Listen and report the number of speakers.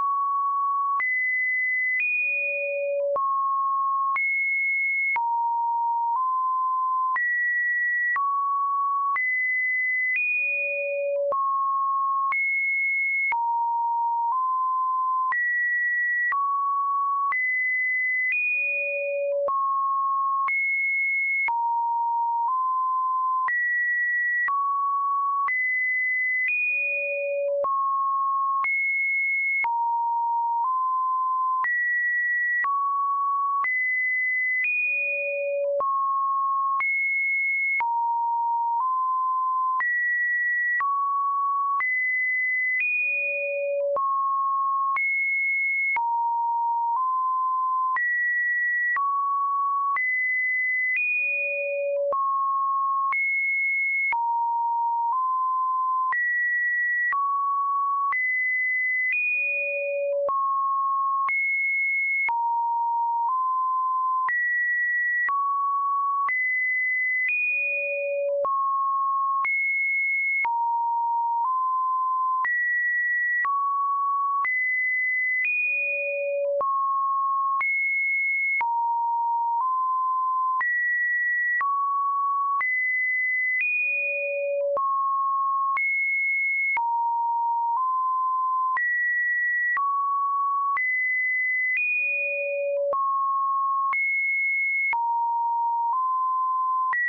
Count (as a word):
zero